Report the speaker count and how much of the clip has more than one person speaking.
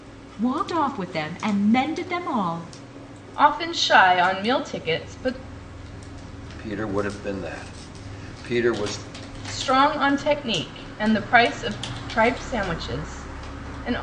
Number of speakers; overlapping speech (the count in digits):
3, no overlap